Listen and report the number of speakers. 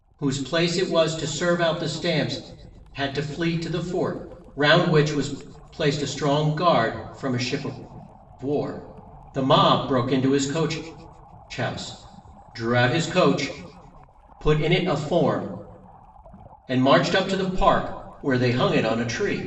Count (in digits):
1